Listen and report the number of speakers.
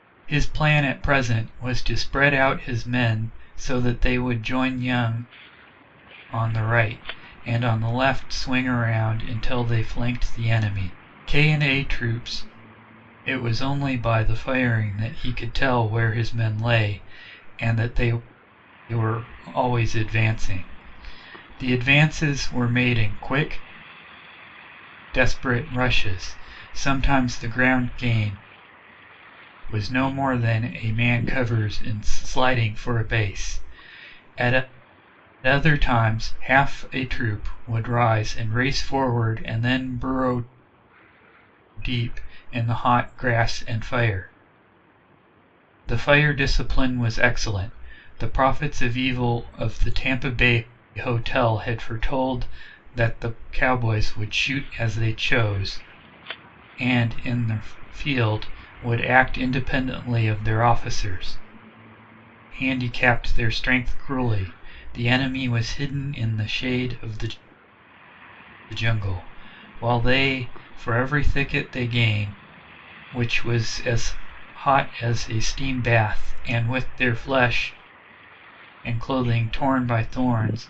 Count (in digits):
1